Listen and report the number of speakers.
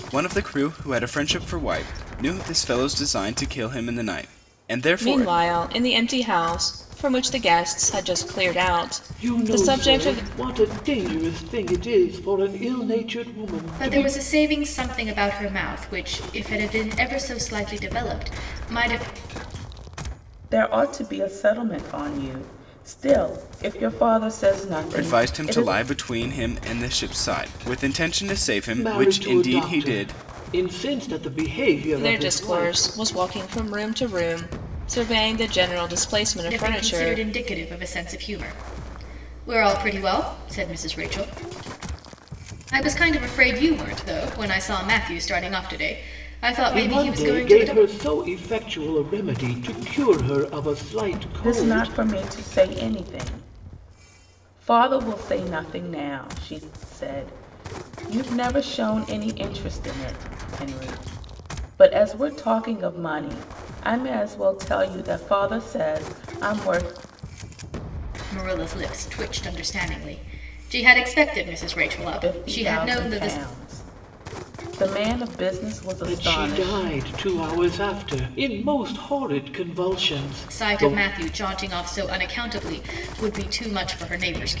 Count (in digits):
5